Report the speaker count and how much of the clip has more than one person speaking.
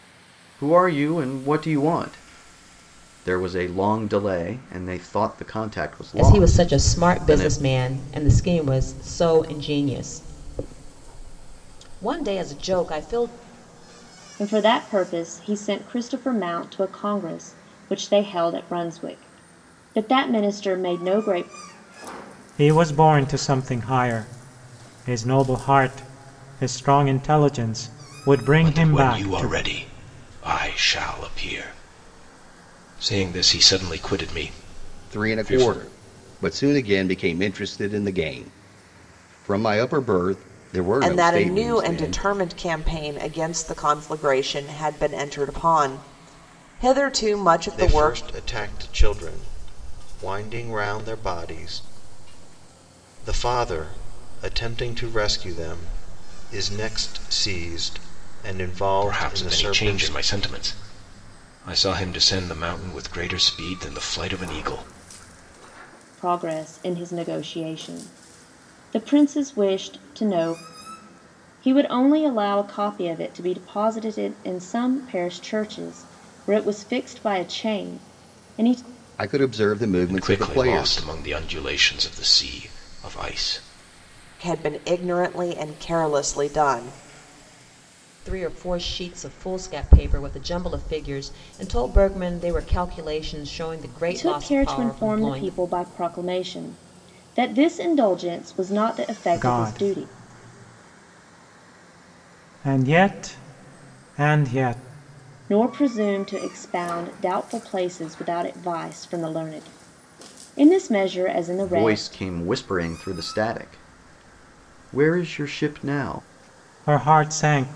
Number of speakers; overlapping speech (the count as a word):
eight, about 9%